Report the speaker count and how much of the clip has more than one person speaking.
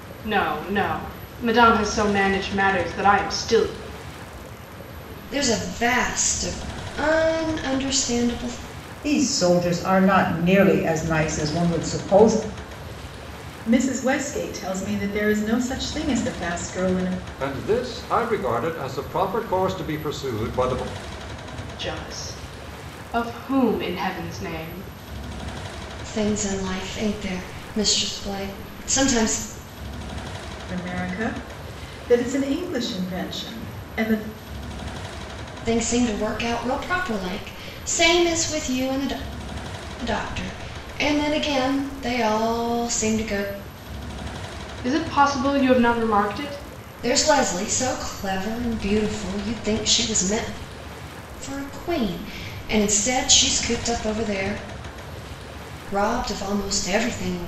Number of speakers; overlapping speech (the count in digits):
5, no overlap